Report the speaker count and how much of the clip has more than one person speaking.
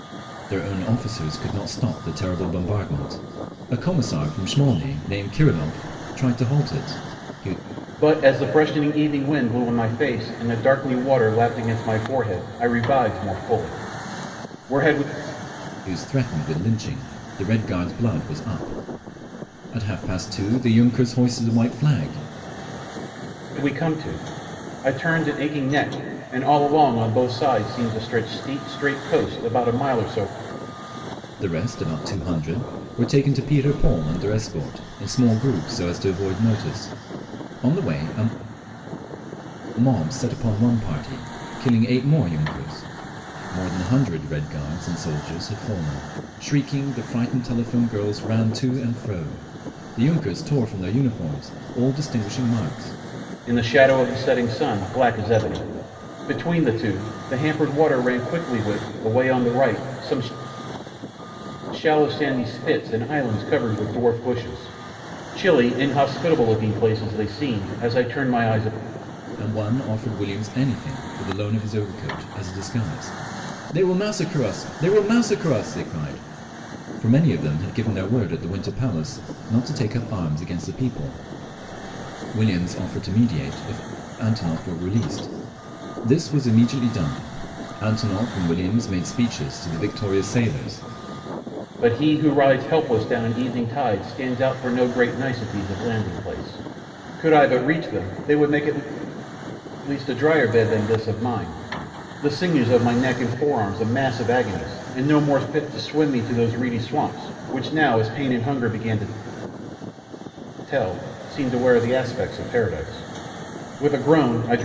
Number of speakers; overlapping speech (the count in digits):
2, no overlap